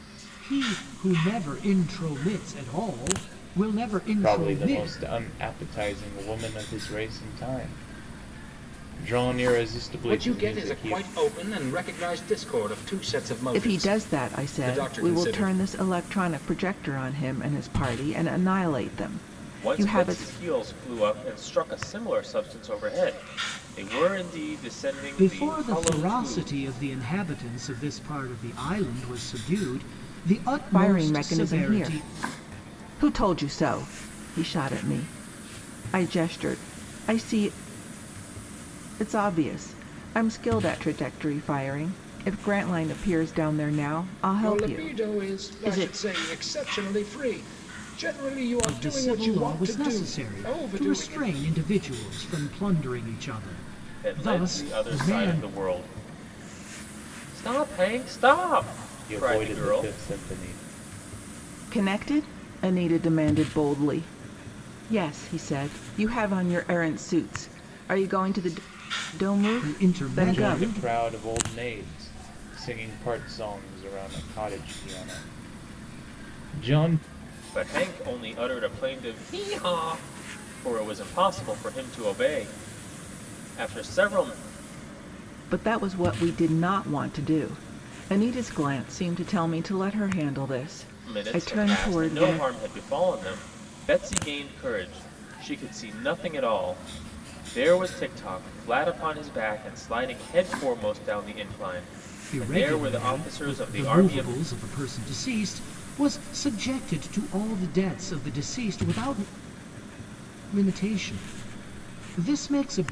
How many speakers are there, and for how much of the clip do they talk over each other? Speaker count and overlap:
five, about 17%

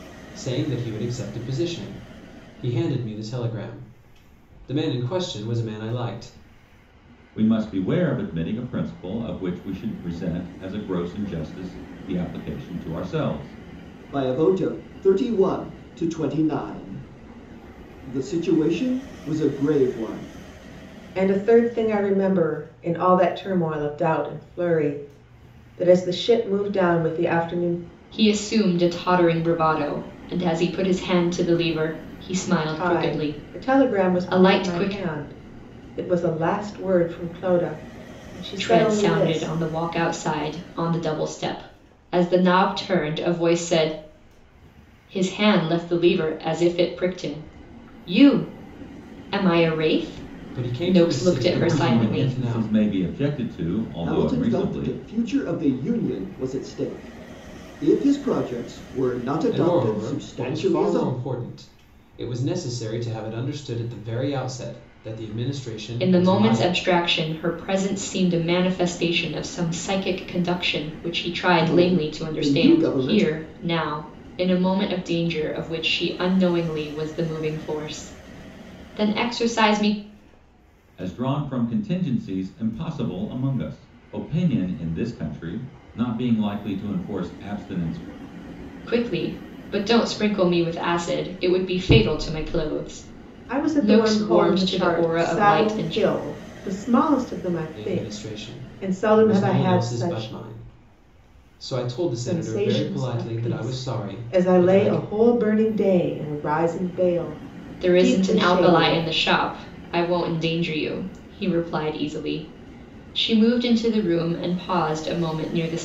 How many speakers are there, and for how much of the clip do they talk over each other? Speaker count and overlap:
five, about 17%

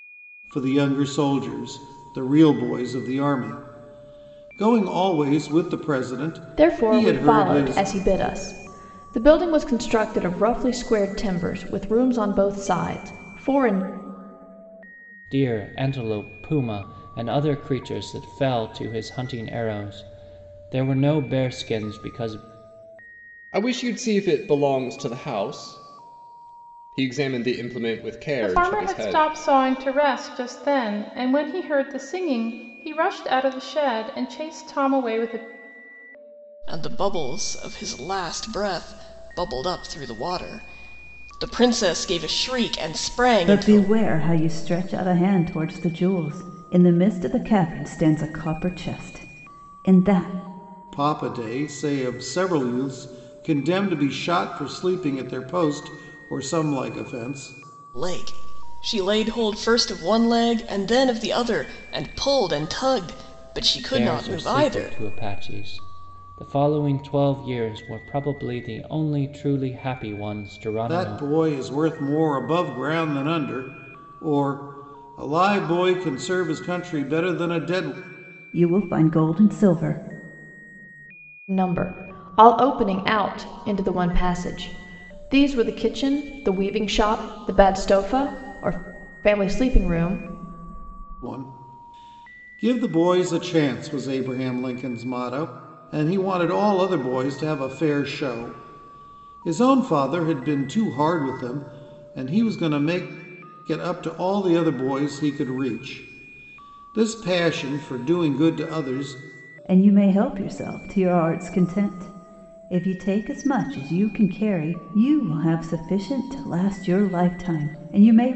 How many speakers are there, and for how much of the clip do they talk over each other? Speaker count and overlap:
seven, about 4%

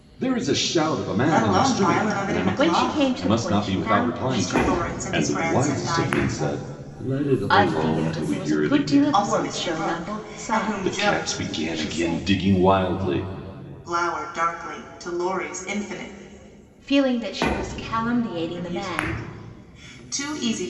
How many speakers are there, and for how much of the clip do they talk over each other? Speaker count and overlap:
three, about 56%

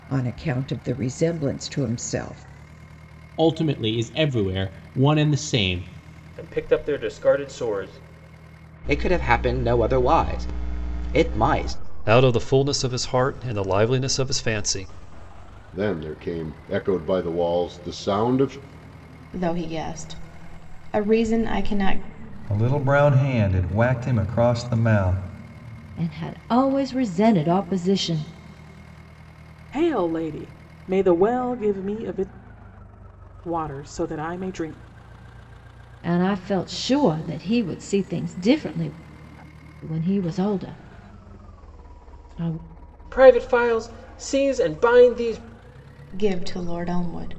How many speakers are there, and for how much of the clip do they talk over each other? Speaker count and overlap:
ten, no overlap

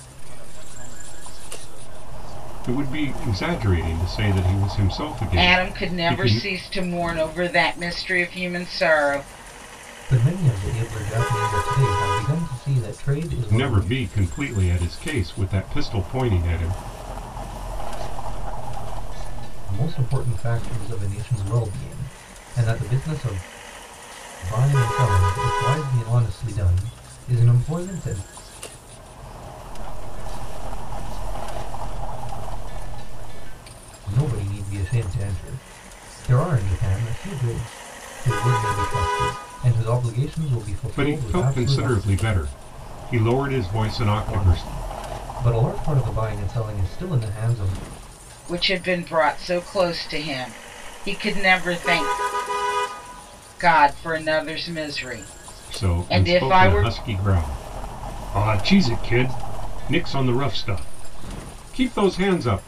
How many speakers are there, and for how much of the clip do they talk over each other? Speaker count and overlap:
four, about 14%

